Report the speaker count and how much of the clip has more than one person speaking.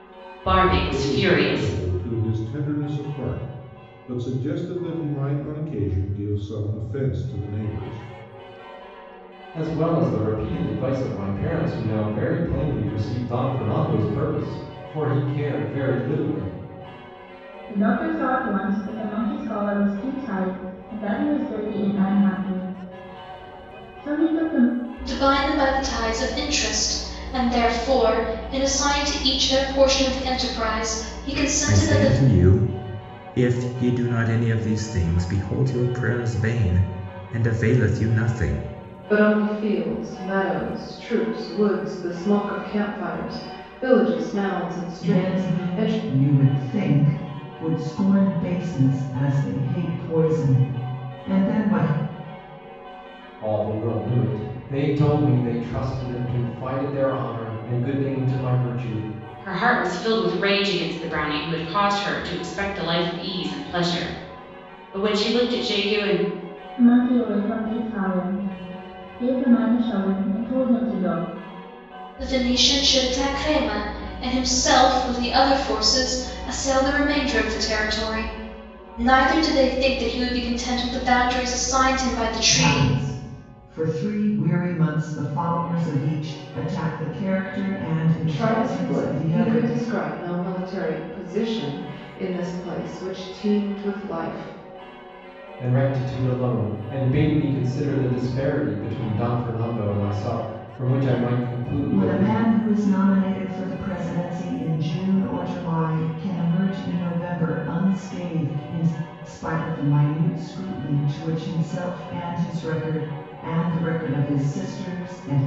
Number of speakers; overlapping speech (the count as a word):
eight, about 4%